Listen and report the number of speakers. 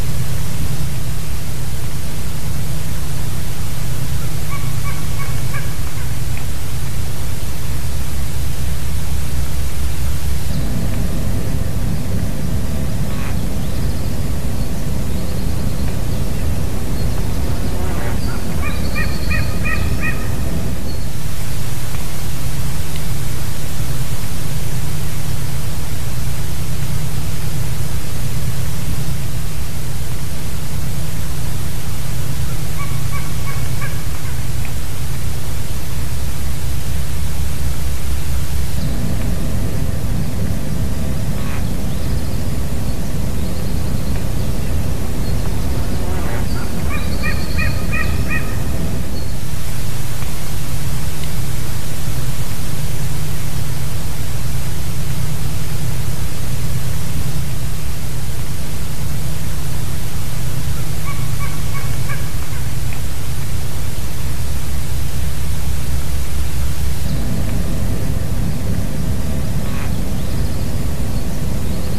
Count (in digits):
0